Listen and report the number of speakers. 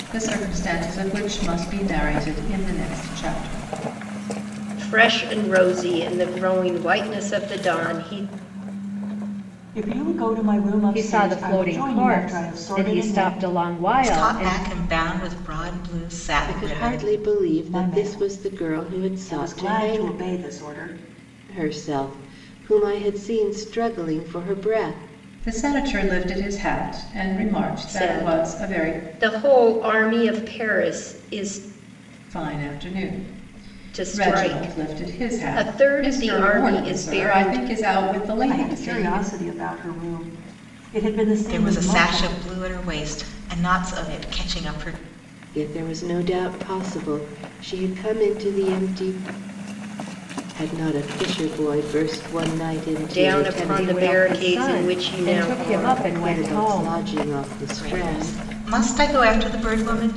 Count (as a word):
six